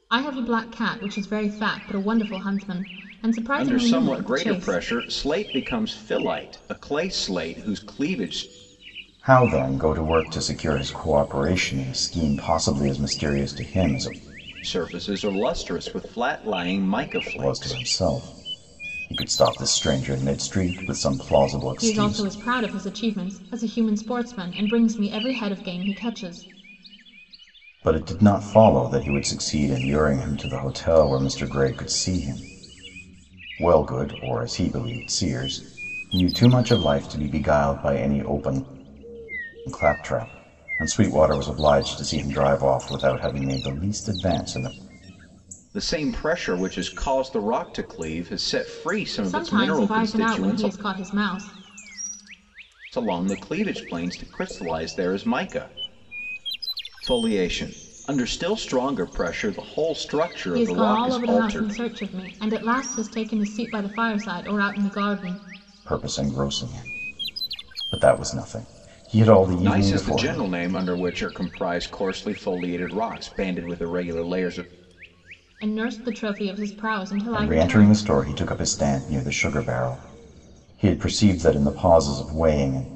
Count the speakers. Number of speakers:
3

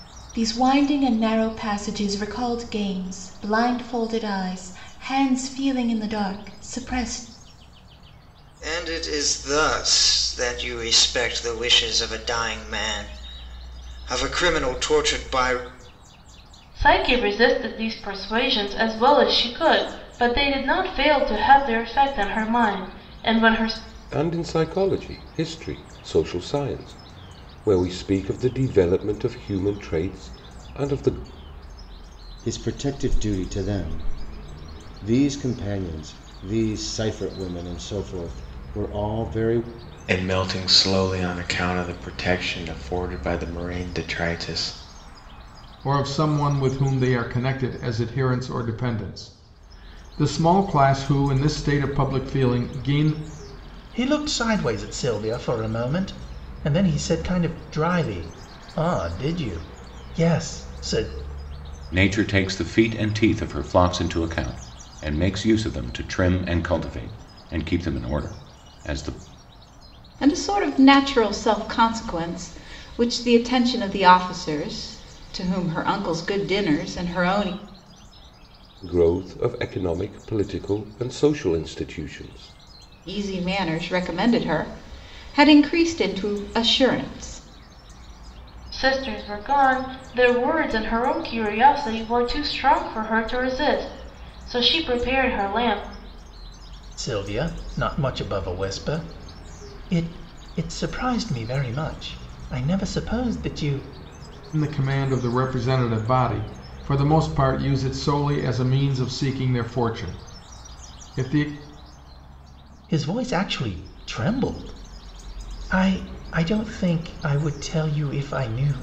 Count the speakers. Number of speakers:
10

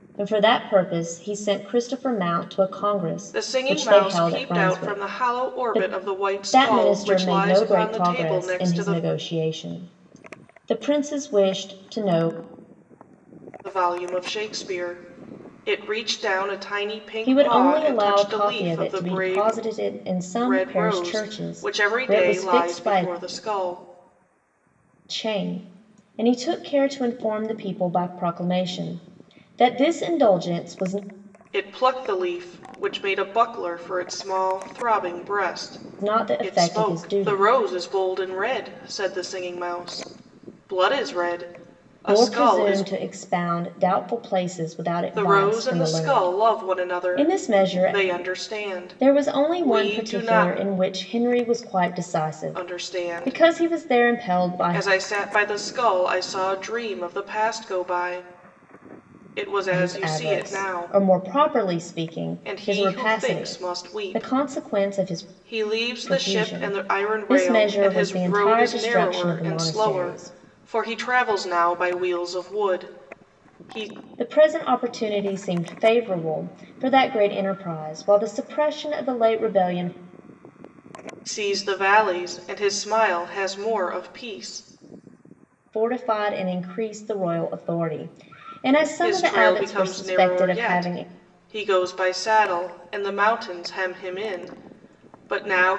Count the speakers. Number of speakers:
2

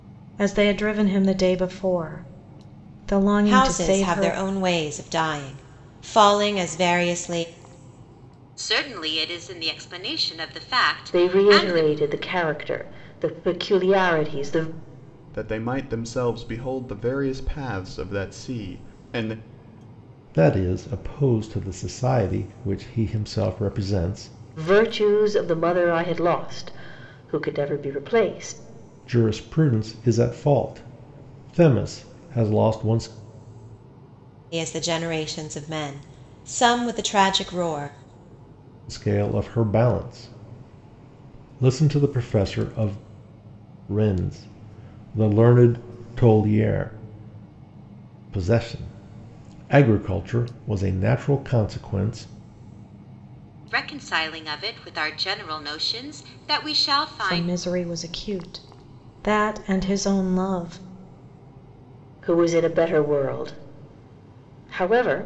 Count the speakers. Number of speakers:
6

